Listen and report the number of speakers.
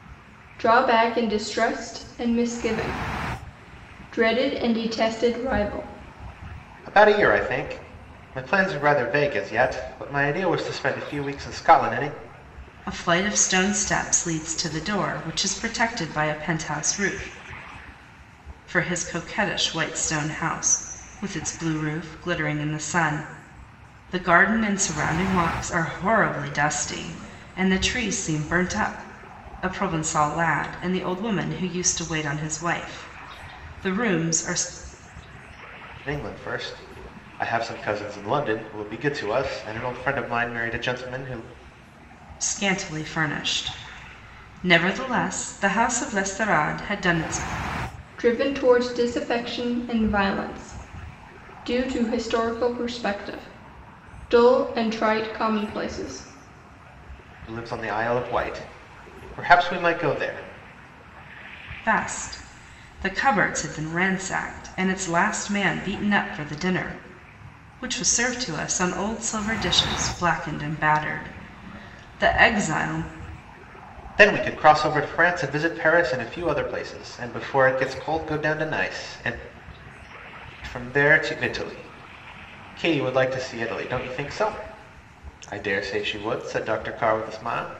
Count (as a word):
three